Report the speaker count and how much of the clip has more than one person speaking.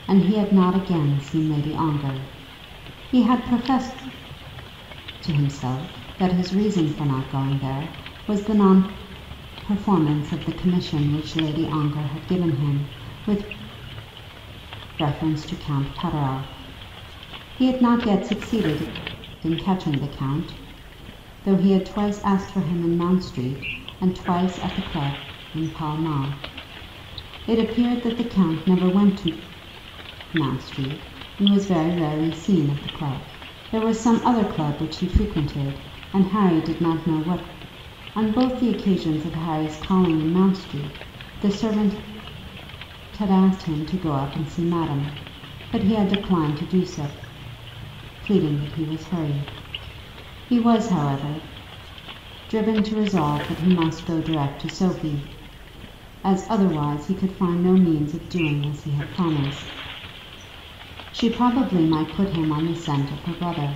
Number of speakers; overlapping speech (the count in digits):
1, no overlap